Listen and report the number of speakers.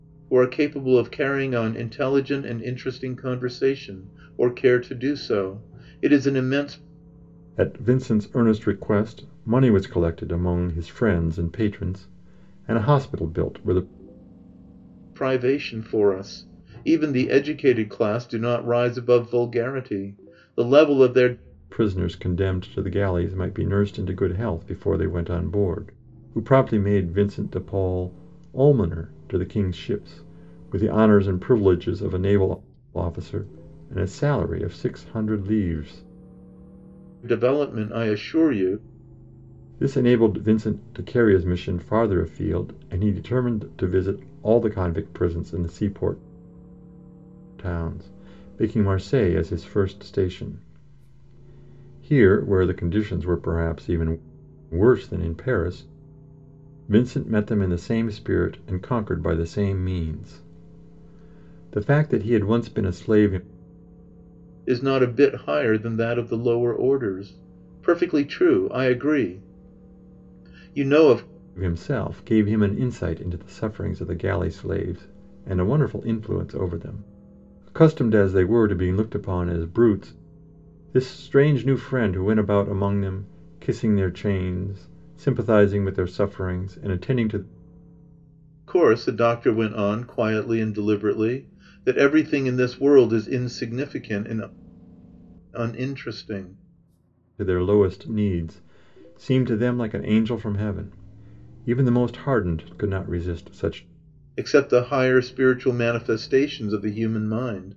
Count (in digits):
2